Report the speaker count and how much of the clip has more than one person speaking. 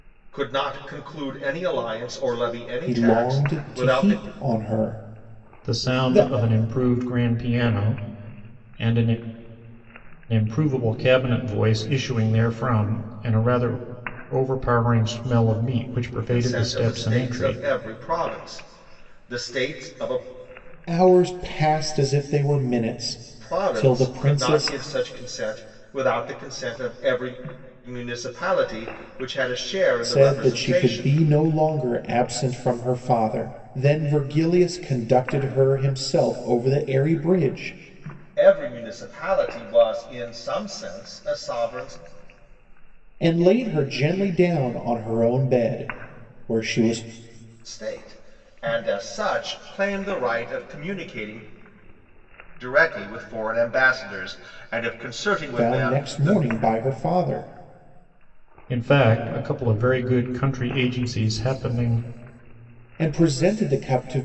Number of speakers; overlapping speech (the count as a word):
three, about 11%